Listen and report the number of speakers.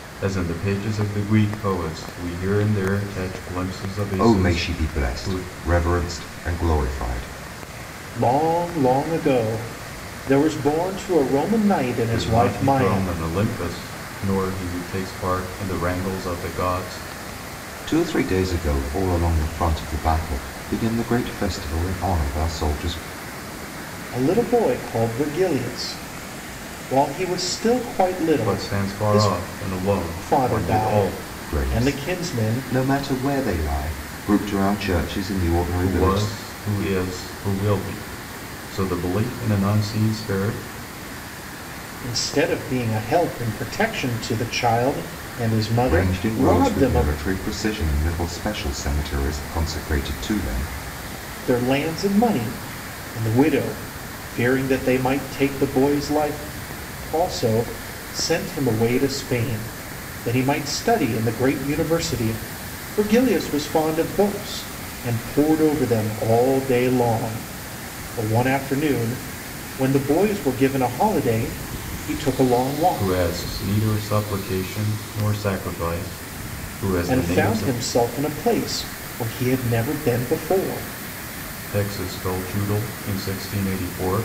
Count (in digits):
3